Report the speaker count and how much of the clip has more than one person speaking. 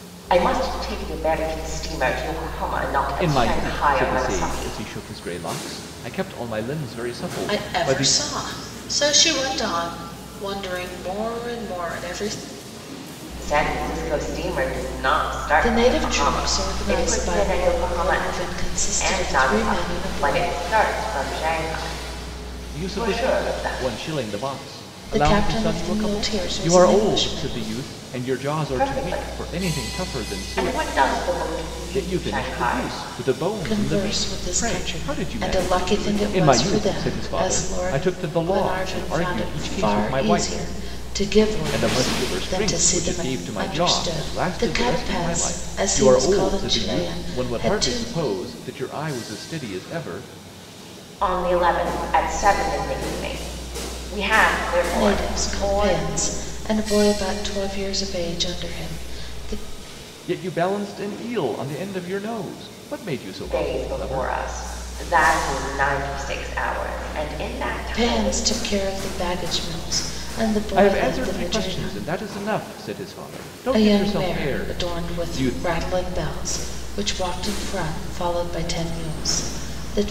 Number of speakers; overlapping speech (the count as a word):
three, about 39%